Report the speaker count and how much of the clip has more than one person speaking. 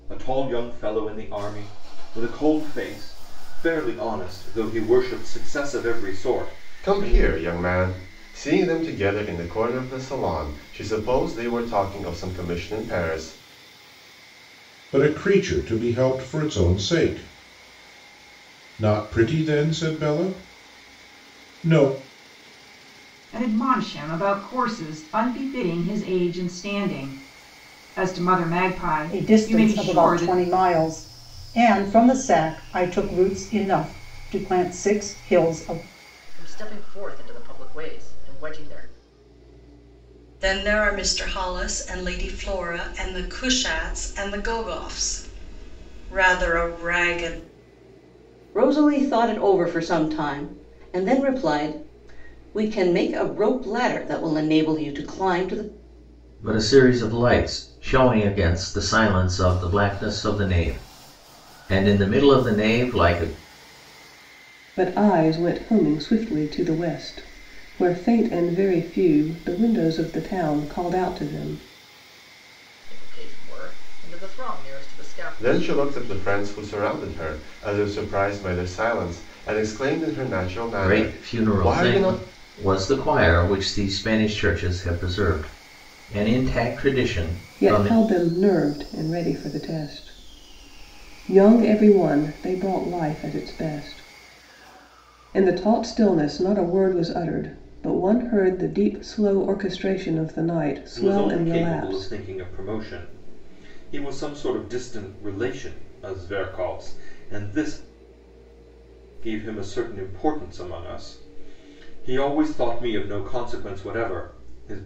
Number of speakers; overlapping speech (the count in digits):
10, about 5%